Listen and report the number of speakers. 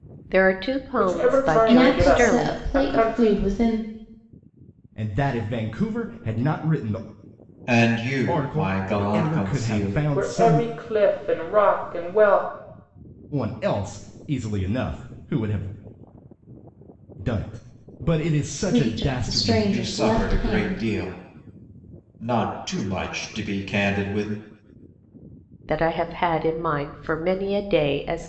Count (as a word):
five